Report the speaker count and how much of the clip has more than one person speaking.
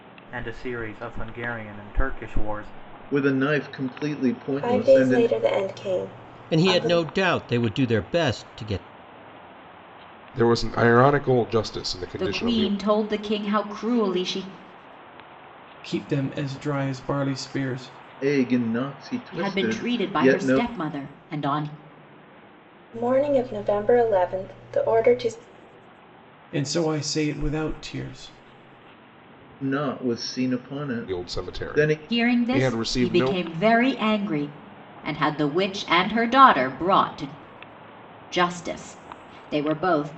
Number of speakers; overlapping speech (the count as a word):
seven, about 14%